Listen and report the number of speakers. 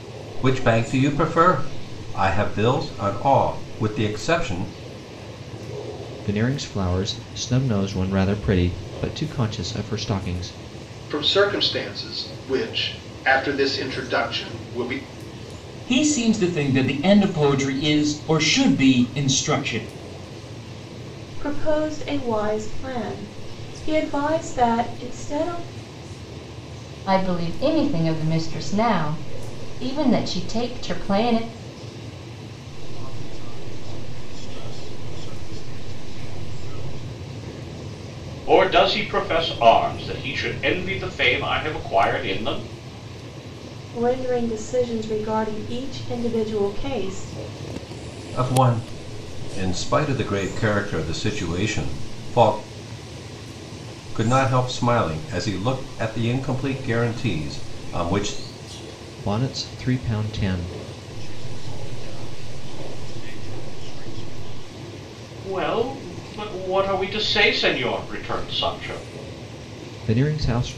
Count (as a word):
eight